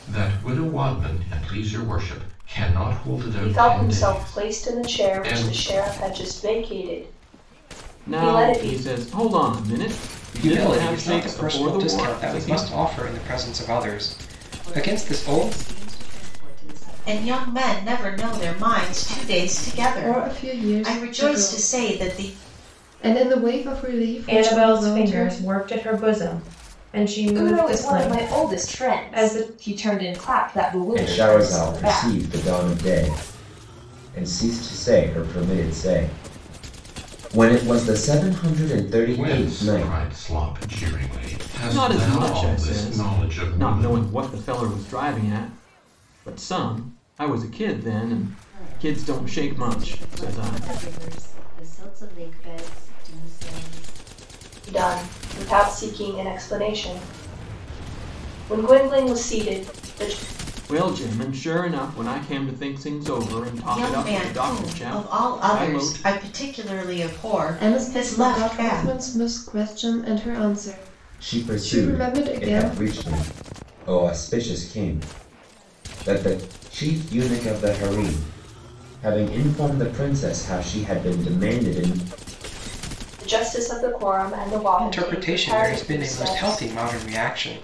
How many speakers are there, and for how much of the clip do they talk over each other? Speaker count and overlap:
10, about 33%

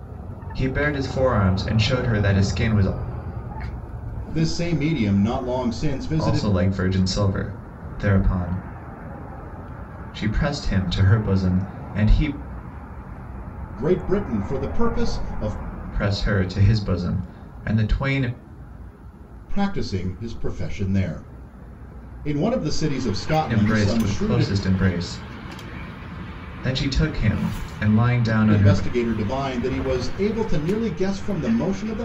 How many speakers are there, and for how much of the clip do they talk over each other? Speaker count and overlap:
2, about 5%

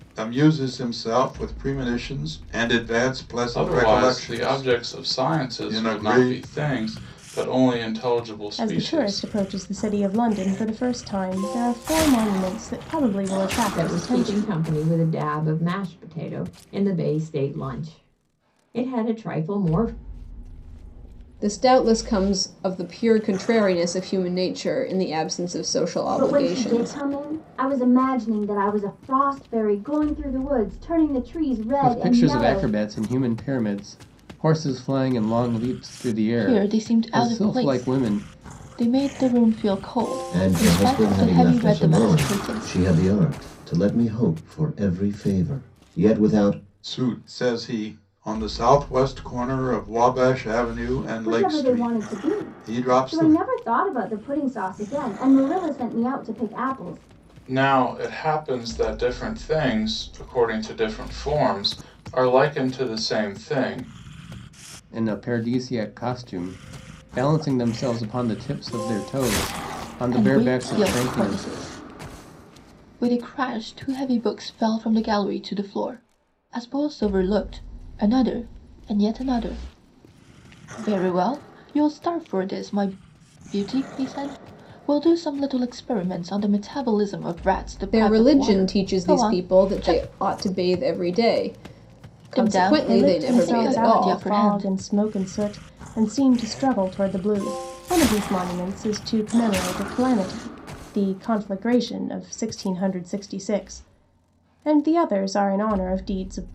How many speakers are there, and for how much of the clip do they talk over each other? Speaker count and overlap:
9, about 18%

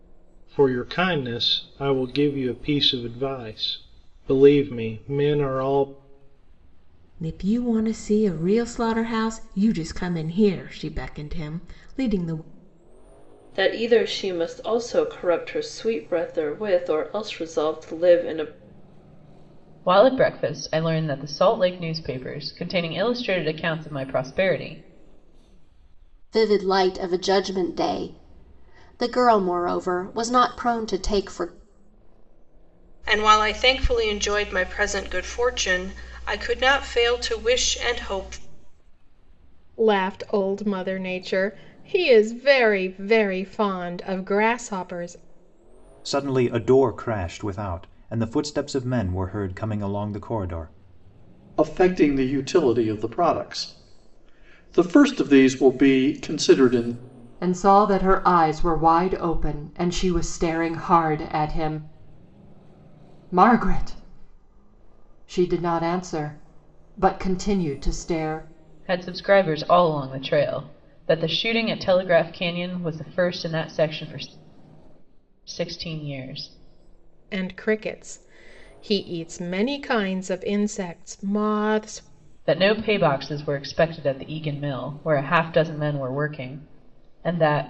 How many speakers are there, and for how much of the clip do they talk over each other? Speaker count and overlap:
10, no overlap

